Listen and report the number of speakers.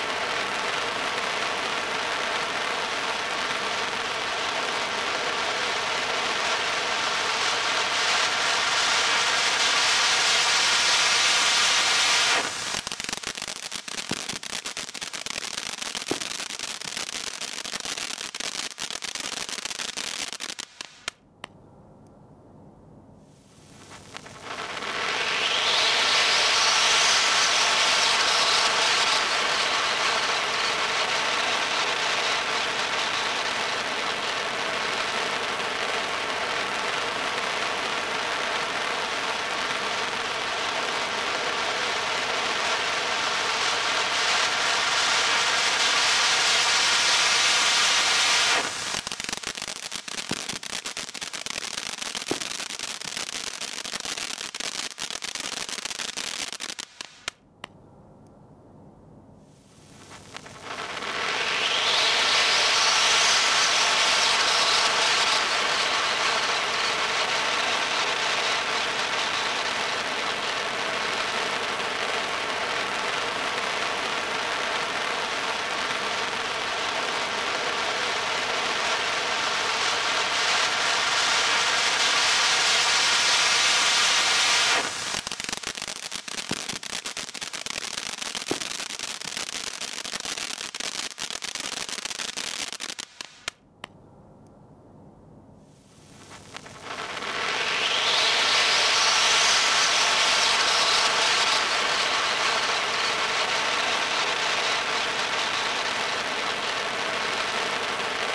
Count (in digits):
0